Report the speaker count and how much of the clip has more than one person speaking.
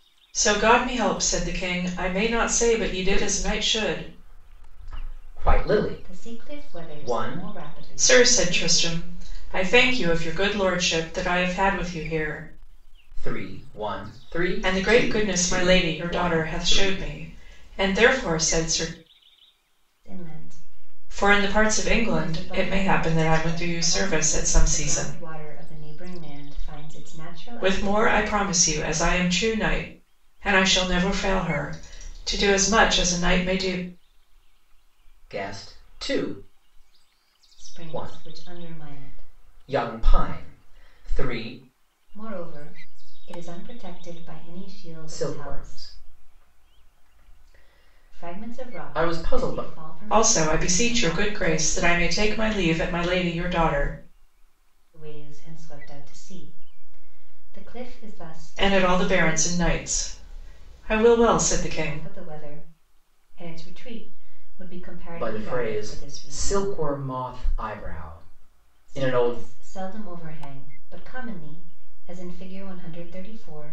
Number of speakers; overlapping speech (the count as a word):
three, about 30%